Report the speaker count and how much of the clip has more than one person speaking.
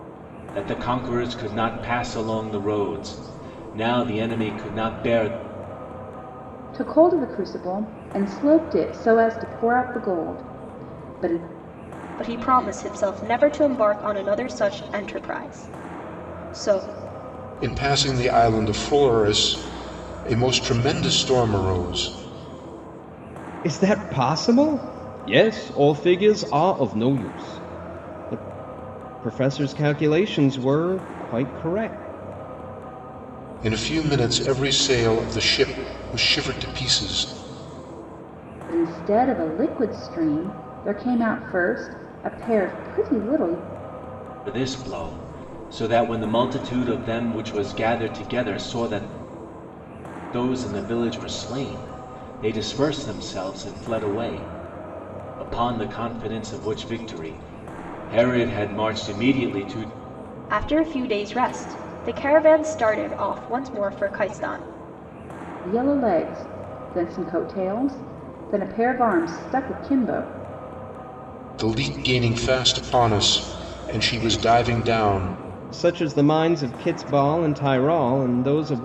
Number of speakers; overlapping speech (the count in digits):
5, no overlap